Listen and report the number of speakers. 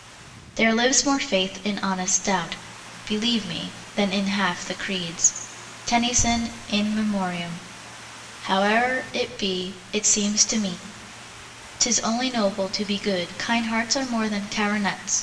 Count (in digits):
1